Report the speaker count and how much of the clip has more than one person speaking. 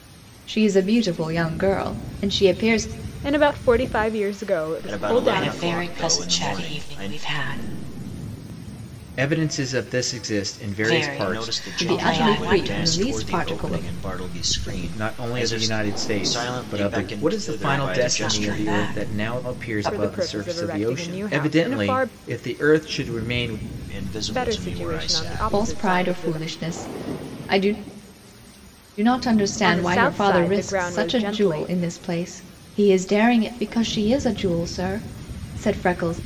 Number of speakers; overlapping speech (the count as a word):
five, about 45%